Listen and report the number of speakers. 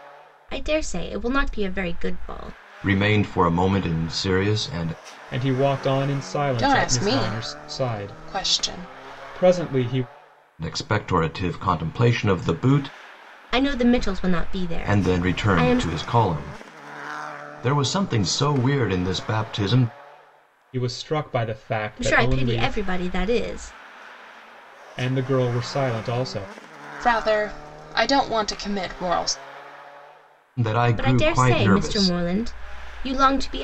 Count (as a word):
four